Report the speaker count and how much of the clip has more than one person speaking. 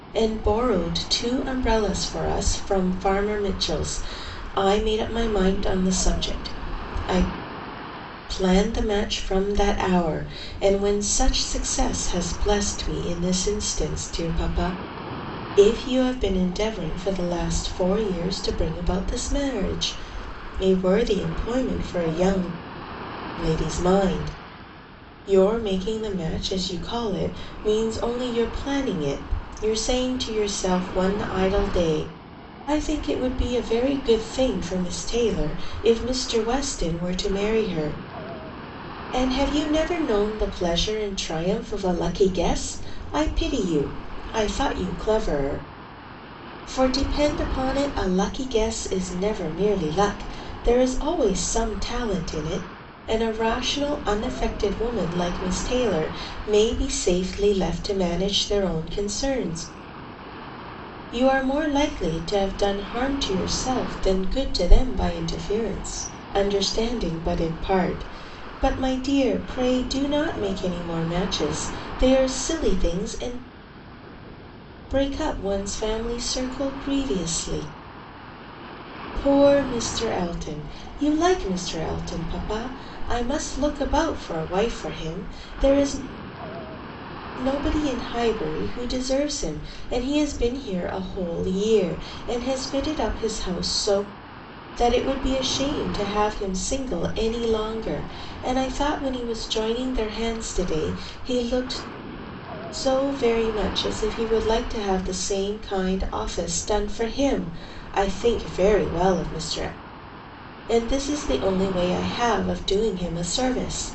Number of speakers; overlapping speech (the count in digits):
1, no overlap